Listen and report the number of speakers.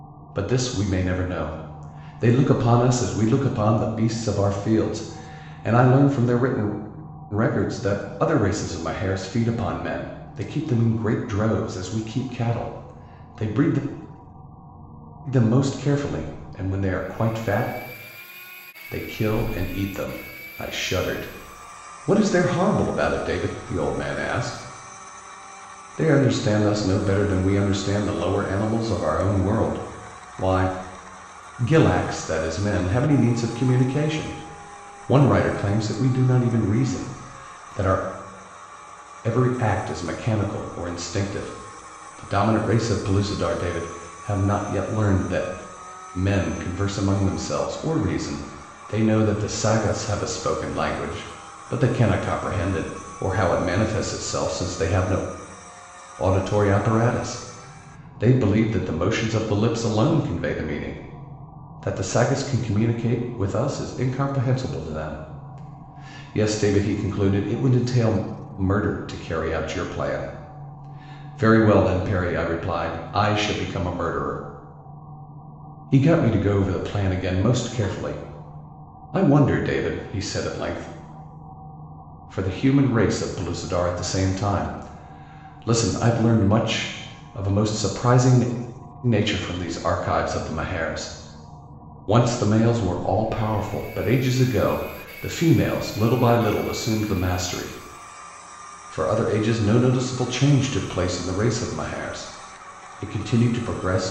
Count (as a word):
one